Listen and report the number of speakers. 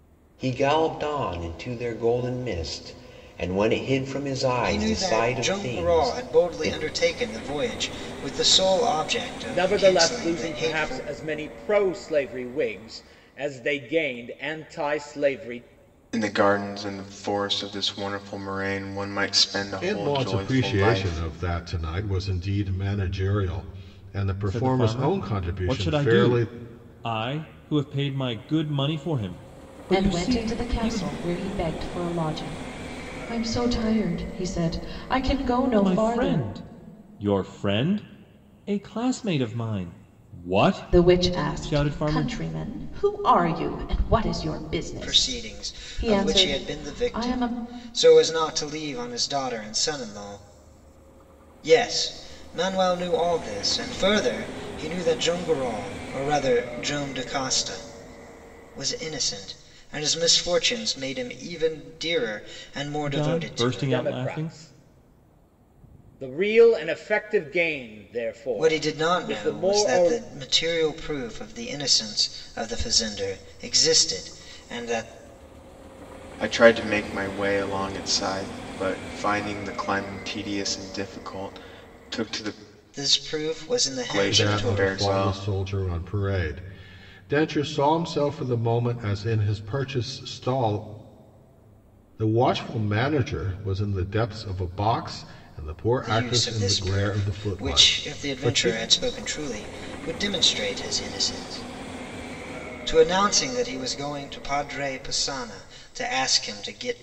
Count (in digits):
7